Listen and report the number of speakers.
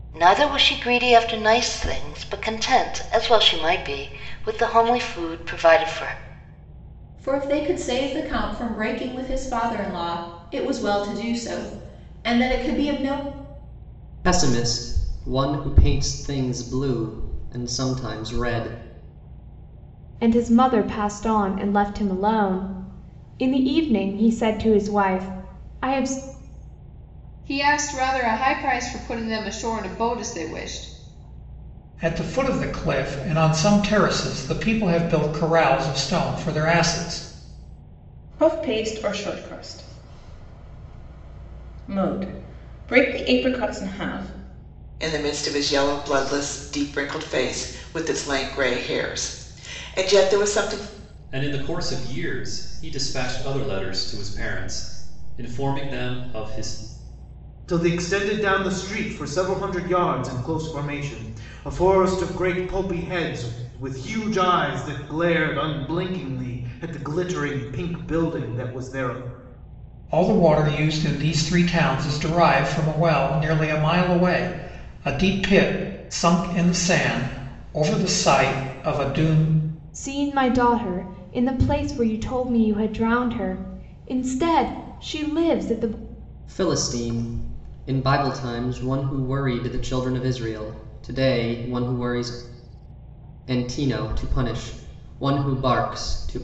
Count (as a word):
ten